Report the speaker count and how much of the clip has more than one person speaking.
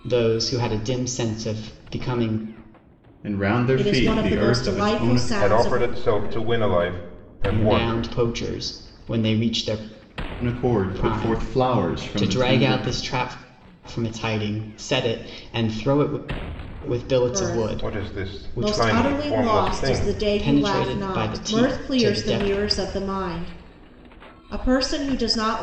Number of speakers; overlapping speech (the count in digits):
5, about 41%